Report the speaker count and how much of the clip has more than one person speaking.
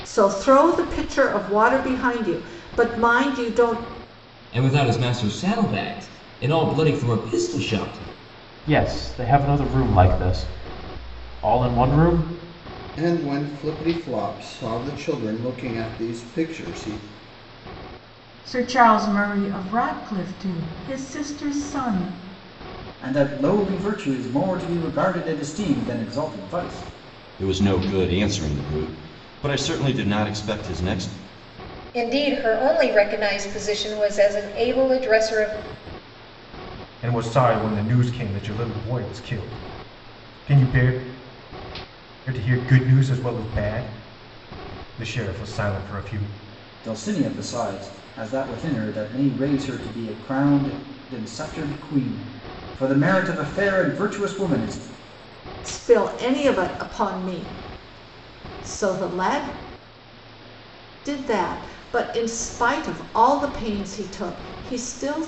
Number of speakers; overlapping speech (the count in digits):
9, no overlap